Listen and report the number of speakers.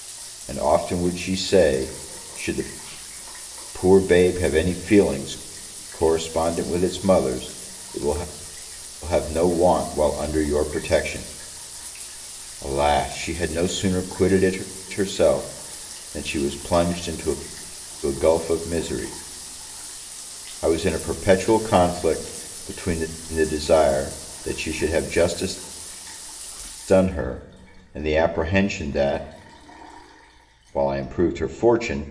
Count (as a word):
one